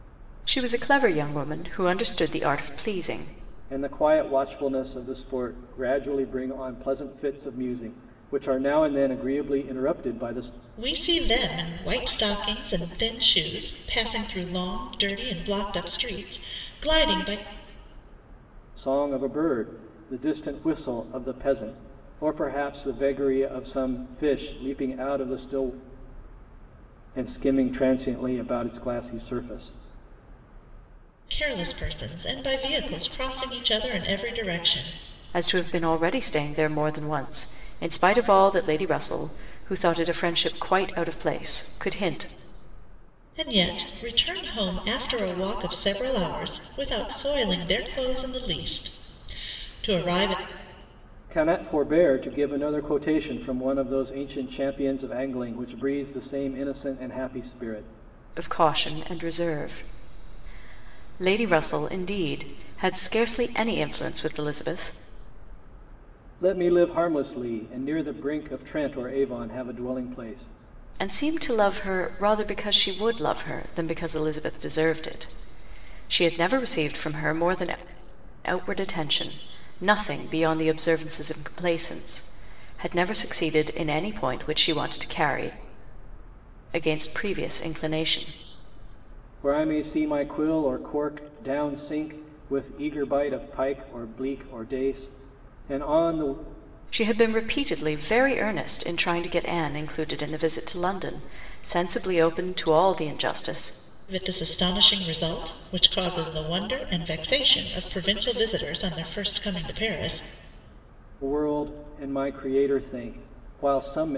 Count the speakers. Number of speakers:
3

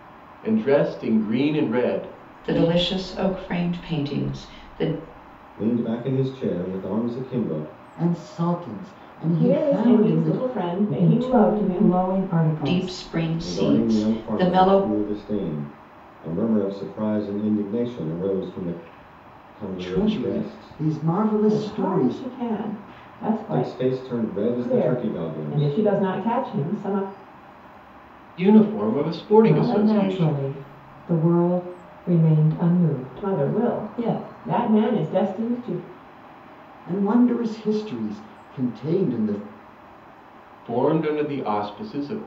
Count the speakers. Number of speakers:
6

